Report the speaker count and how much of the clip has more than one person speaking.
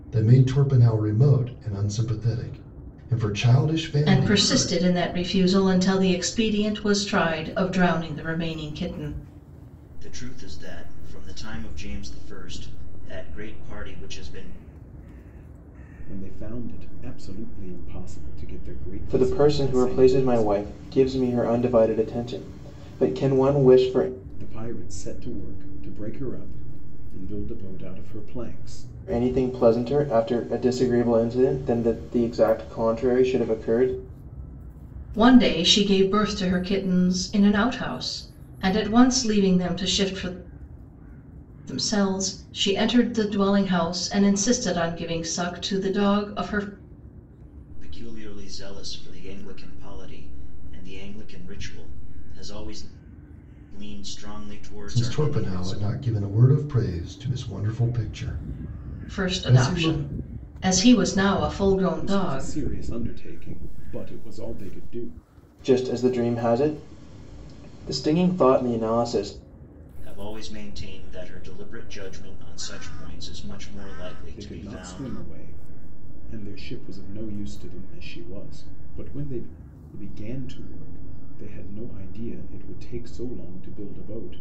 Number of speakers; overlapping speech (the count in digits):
5, about 7%